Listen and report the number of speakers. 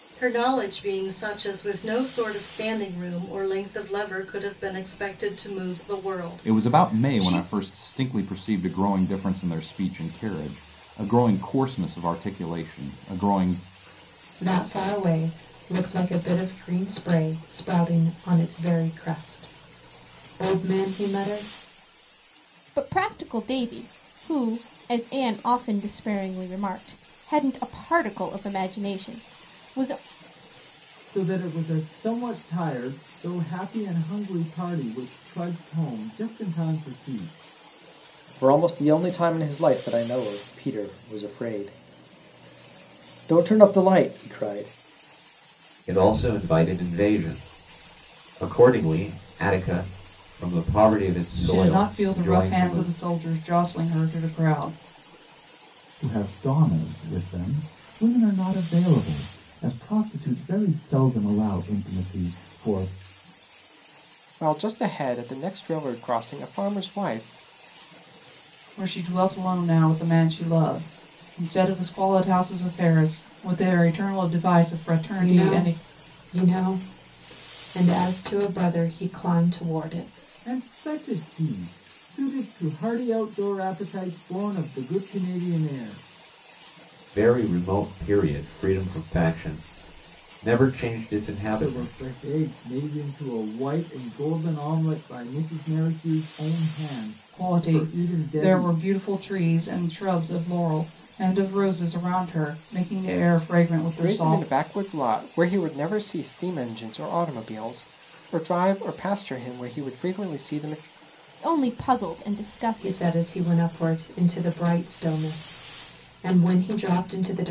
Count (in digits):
10